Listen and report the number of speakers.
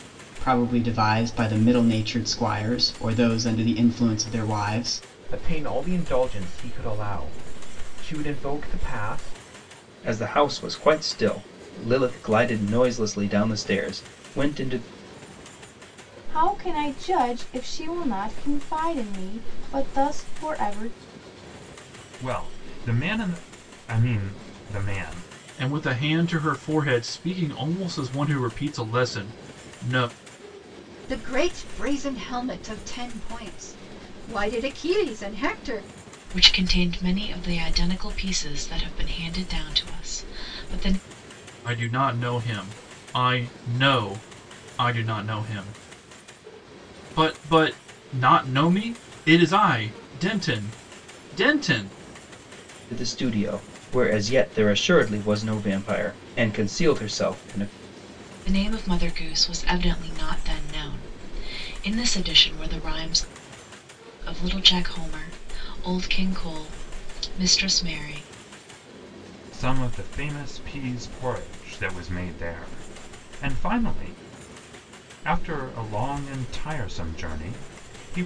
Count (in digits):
8